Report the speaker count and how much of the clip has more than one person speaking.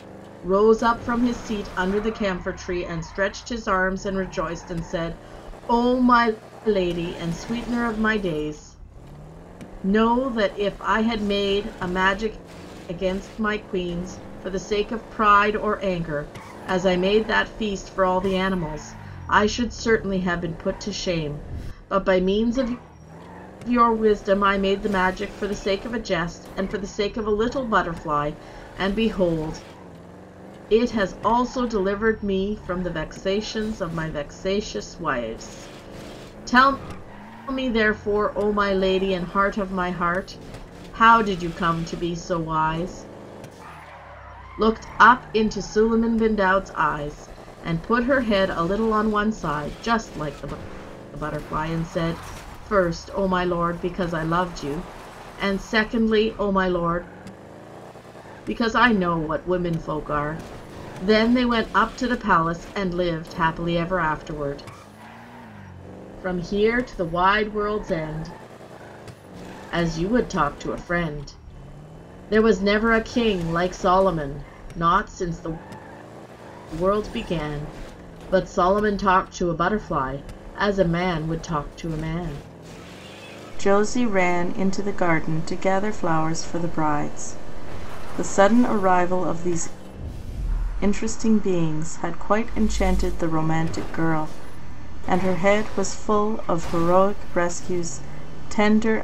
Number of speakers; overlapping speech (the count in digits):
1, no overlap